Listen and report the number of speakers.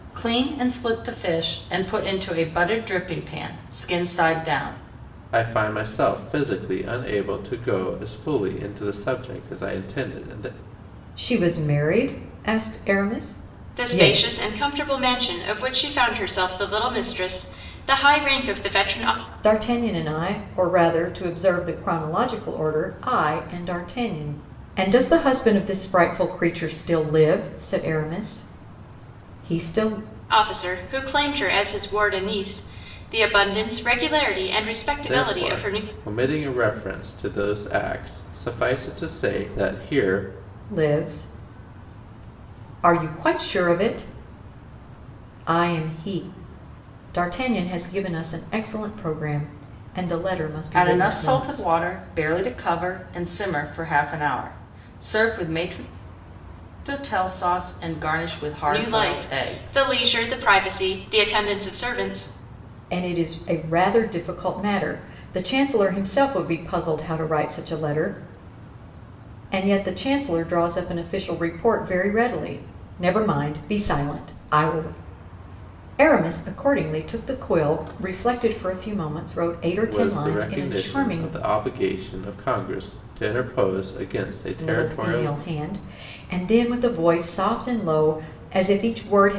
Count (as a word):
four